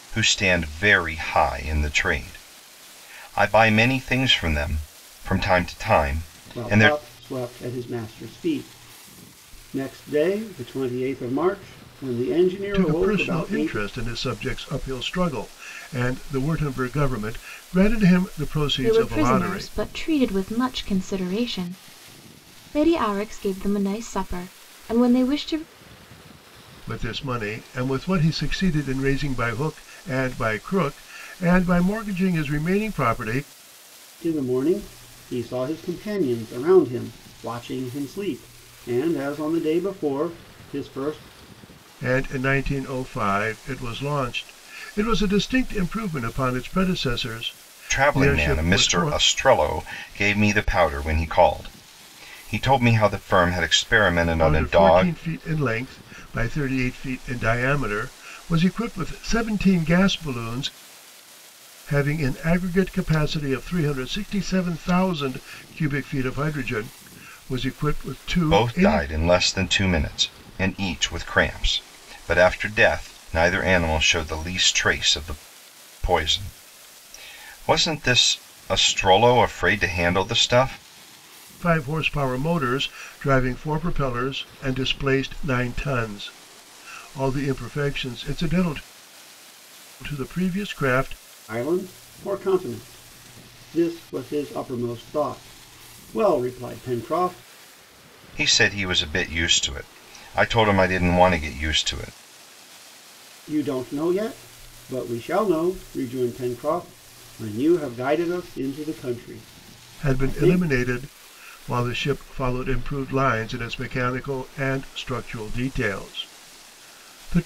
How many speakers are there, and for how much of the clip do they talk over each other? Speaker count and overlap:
4, about 5%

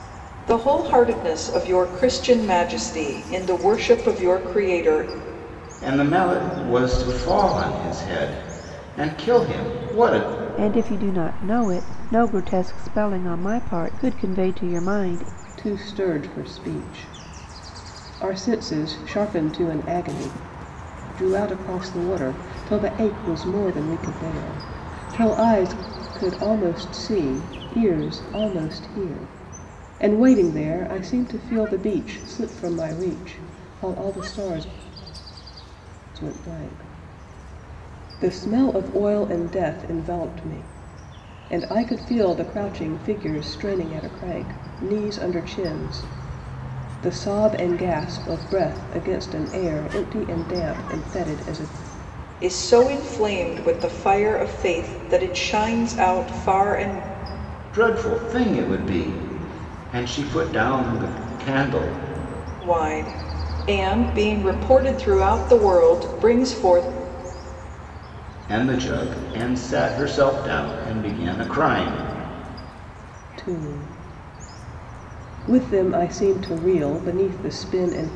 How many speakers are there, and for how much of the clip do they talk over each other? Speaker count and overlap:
4, no overlap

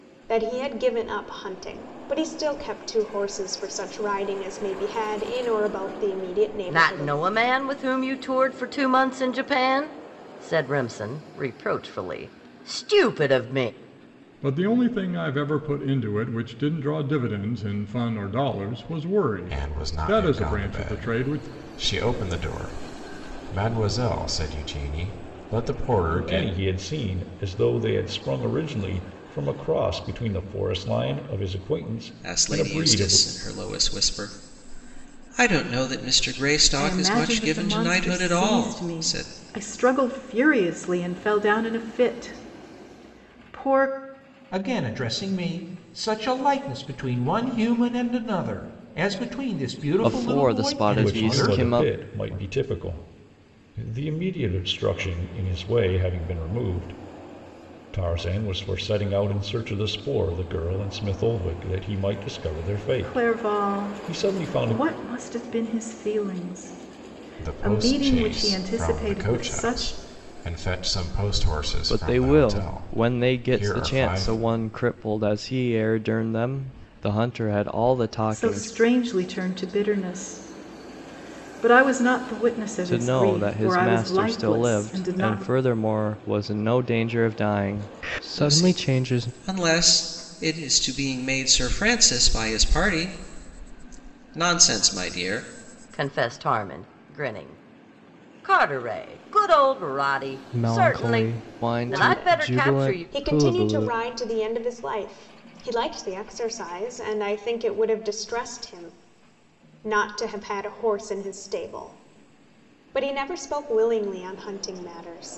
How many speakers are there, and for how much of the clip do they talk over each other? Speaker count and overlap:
9, about 20%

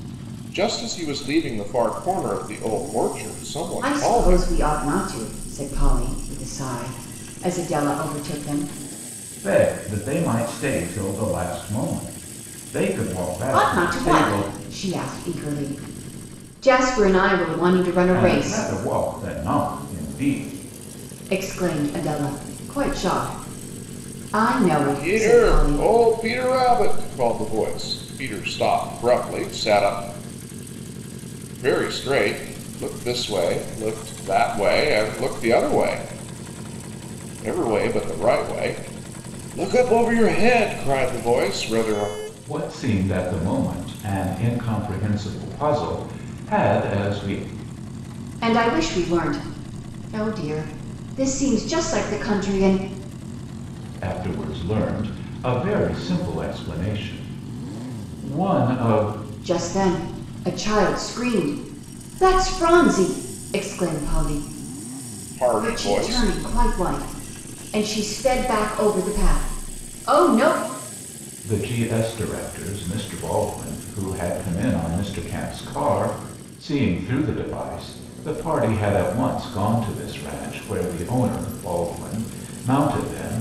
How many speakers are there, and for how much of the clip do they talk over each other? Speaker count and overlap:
3, about 5%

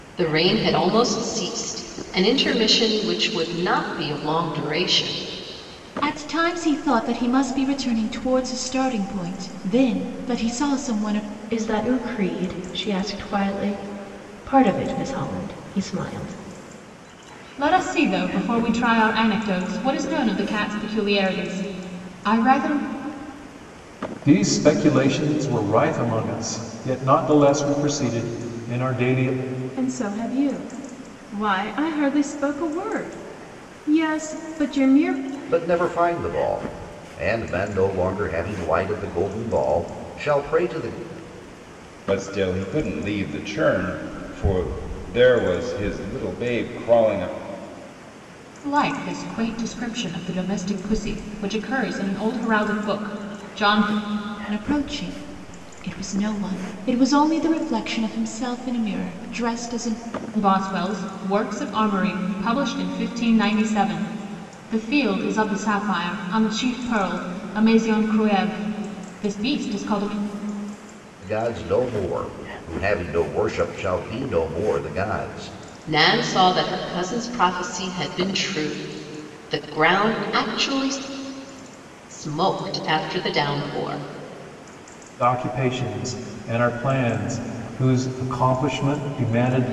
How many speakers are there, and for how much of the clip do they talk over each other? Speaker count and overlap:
8, no overlap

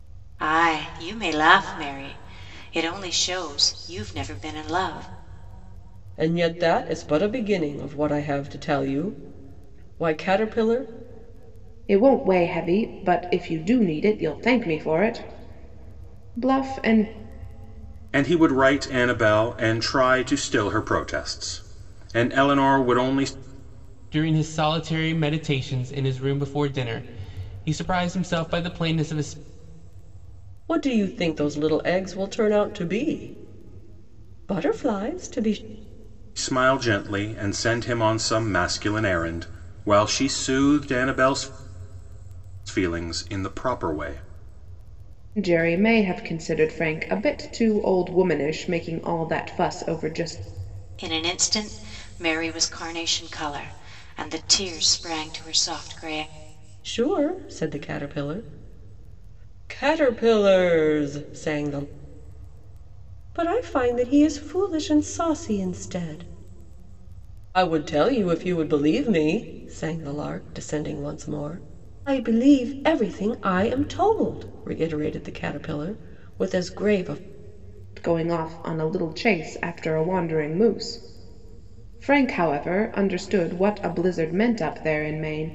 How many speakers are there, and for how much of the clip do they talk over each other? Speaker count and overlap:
5, no overlap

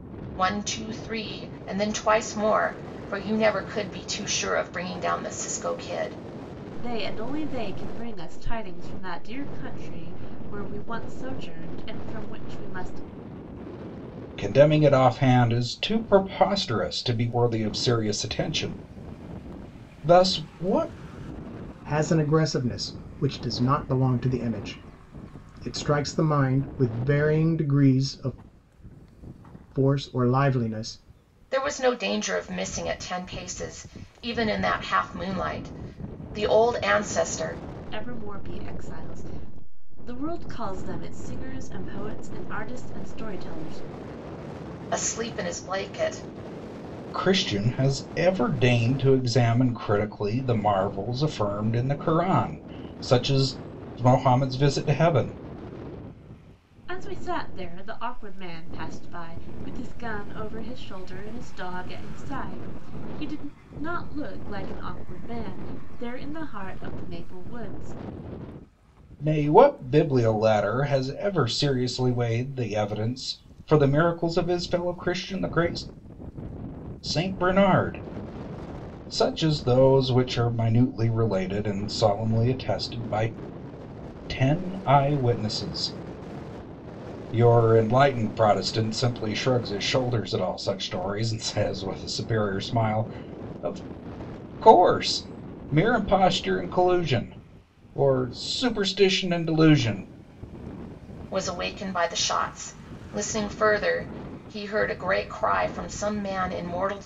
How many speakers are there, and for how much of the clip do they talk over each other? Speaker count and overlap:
4, no overlap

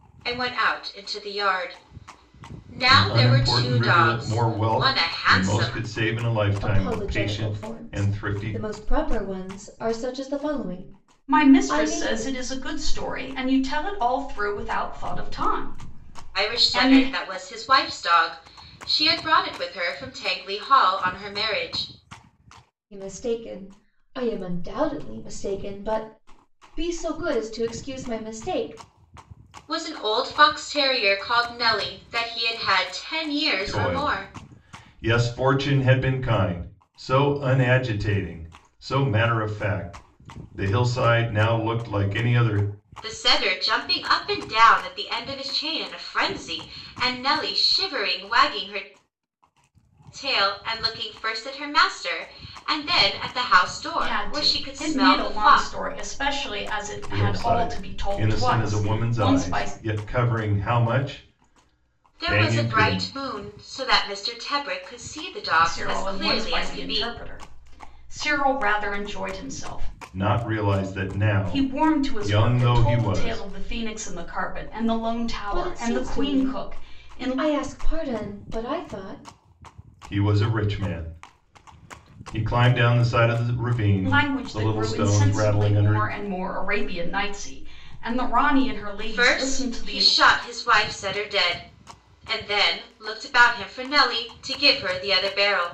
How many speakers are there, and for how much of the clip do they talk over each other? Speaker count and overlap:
4, about 22%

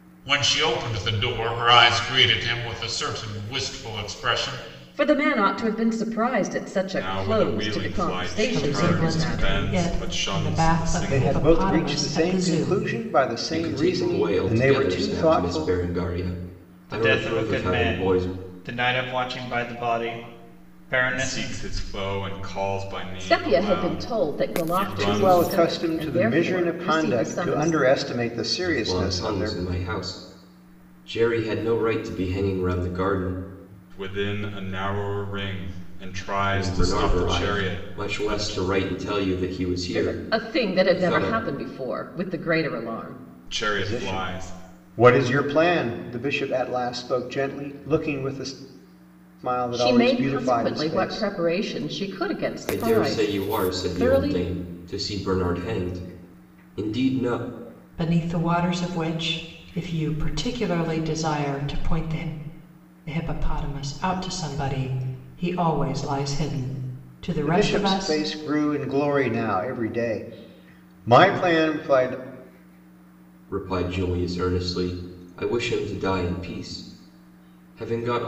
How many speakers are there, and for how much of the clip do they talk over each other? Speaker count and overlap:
7, about 31%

